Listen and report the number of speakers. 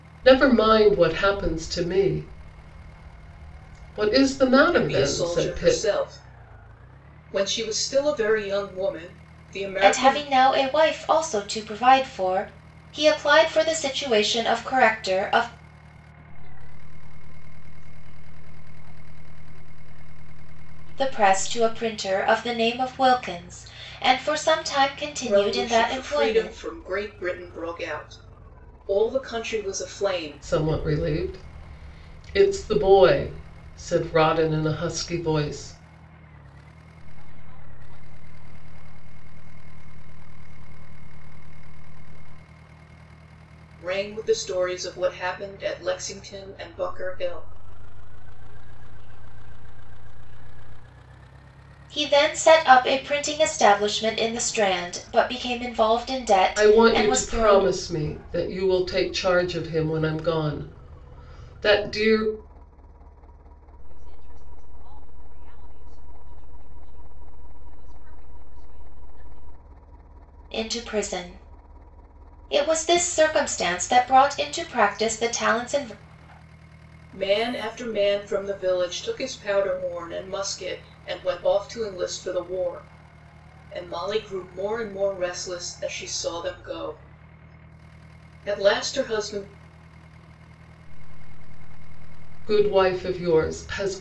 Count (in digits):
4